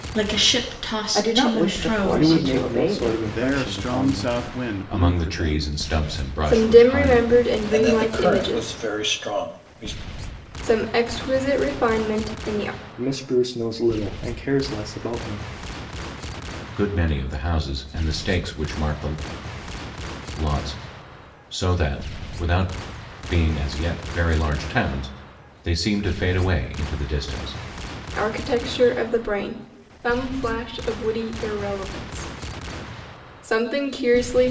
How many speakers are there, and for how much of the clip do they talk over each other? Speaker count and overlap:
7, about 17%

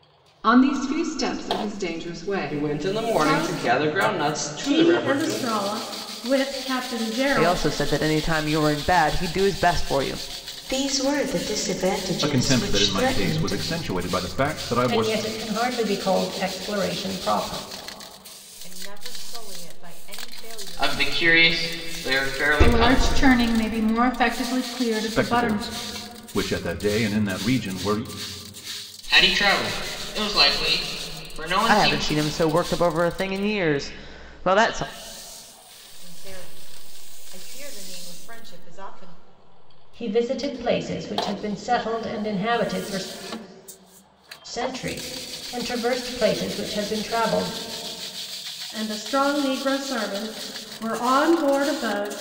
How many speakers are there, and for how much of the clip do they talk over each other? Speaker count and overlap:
10, about 13%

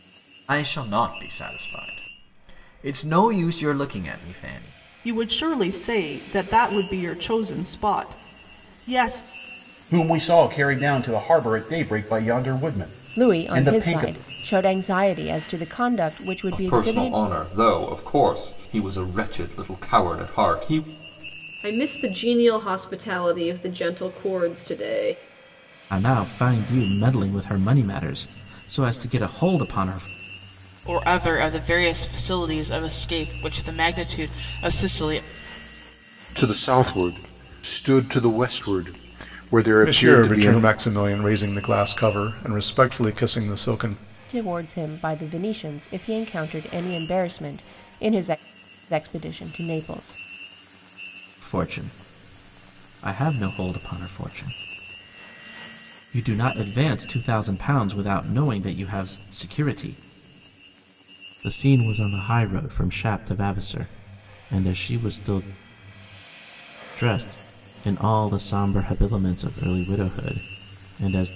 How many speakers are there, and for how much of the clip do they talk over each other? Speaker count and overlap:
10, about 4%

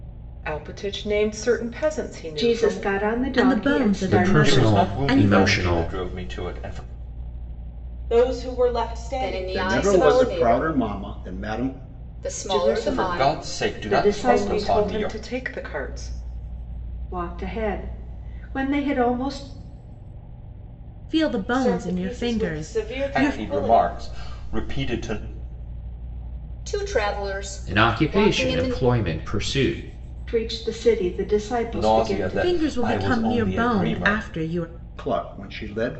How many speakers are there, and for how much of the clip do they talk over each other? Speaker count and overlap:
8, about 37%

